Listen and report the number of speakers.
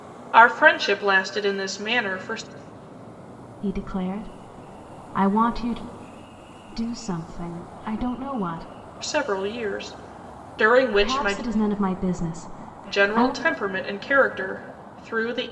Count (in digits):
2